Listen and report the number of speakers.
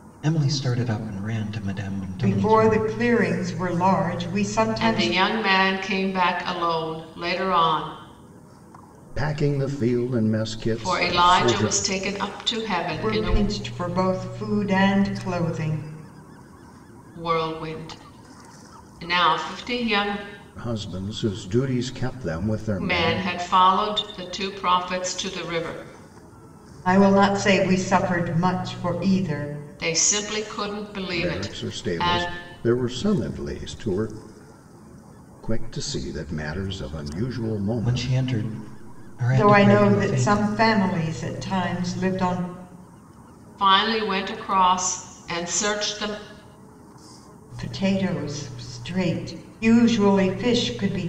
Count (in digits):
4